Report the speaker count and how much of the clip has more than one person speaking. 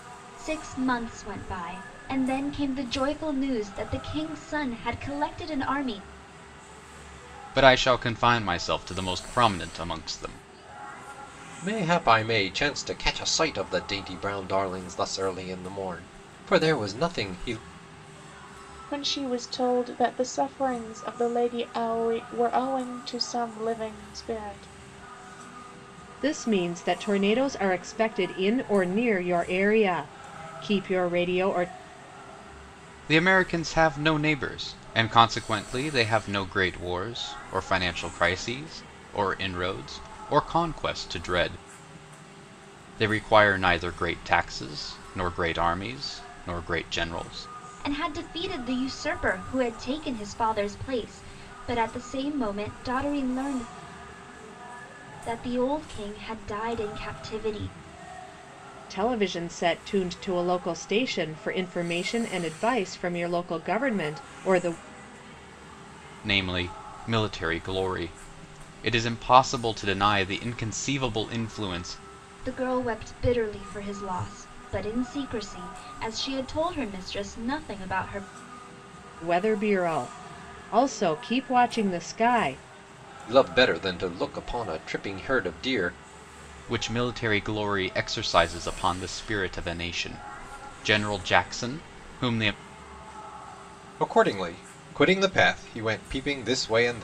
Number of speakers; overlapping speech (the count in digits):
5, no overlap